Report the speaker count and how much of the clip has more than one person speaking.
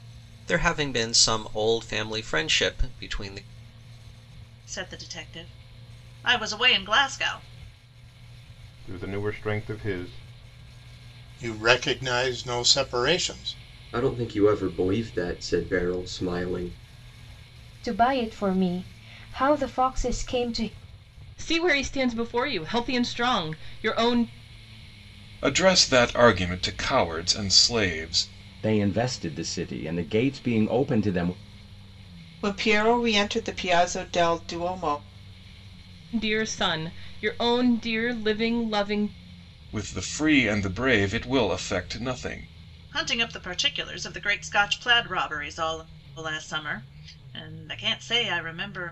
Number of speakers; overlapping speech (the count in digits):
10, no overlap